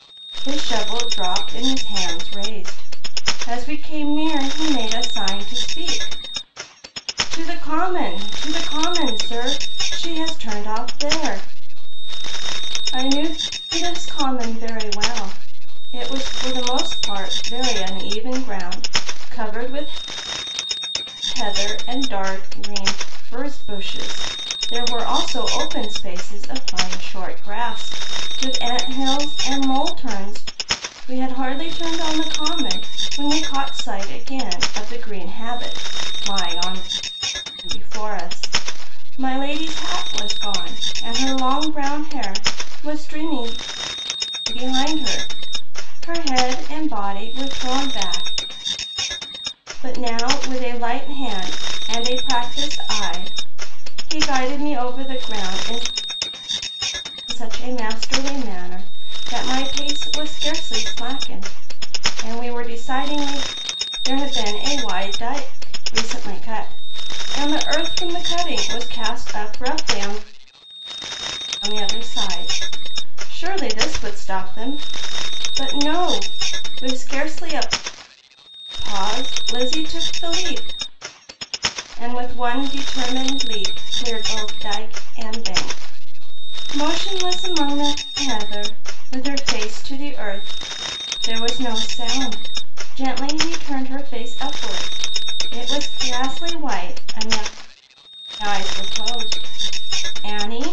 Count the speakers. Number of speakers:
1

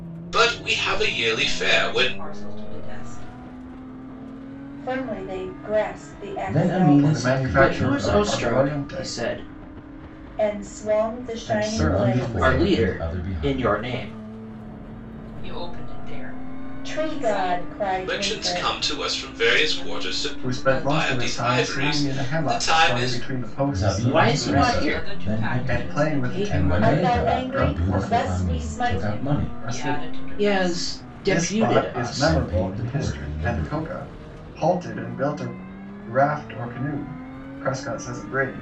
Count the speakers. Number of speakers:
6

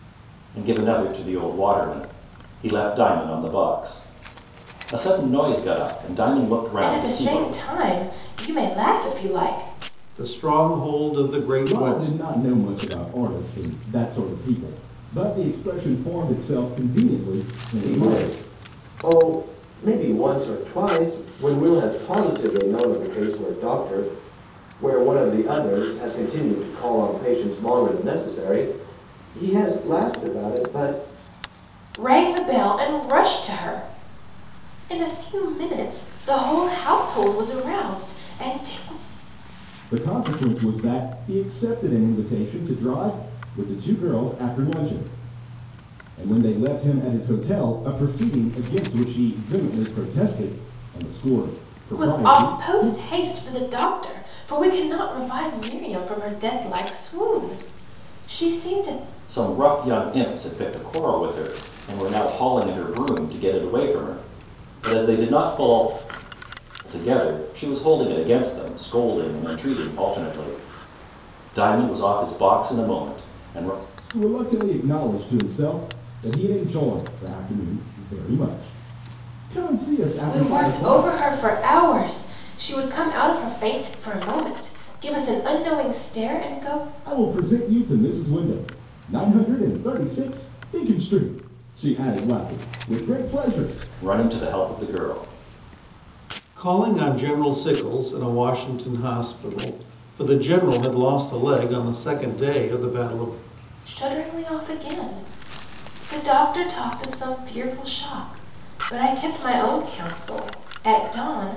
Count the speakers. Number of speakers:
5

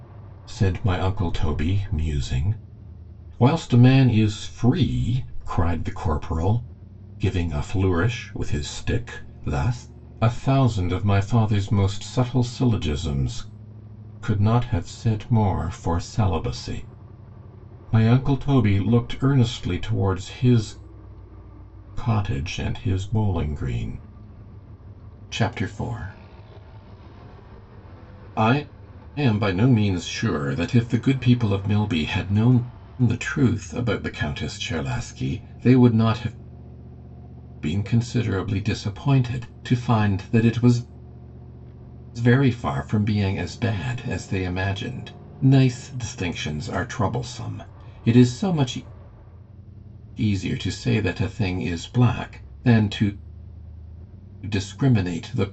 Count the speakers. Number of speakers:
1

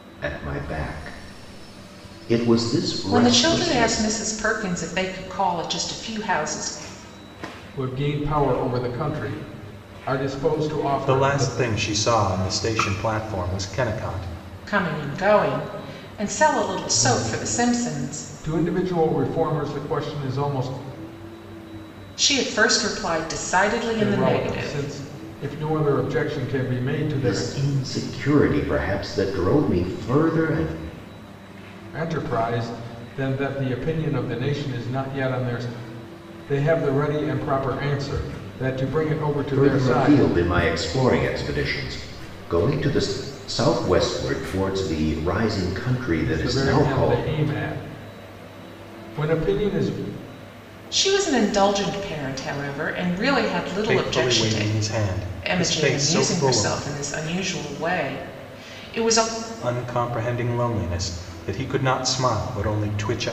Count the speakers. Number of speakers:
4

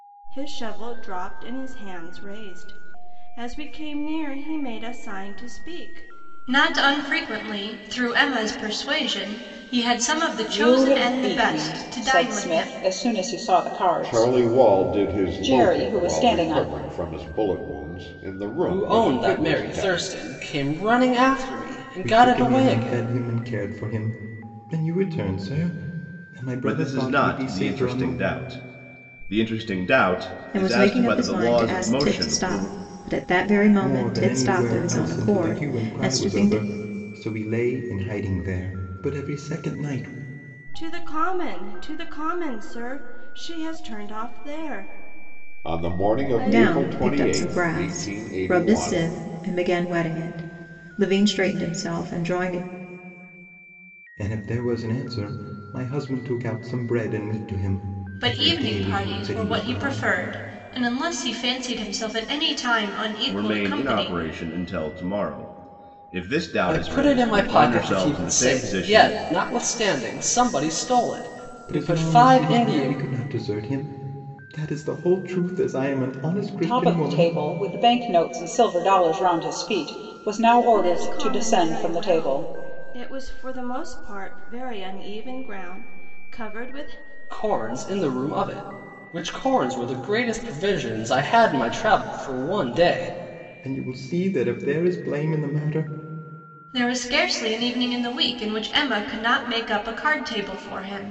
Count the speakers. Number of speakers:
8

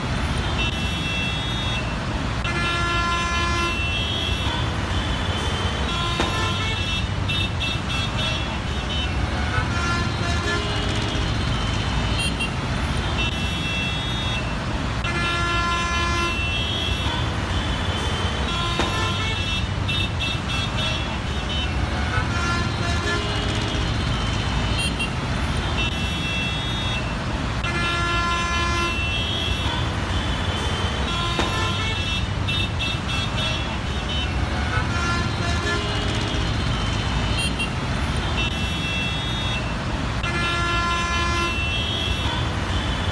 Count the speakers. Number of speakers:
0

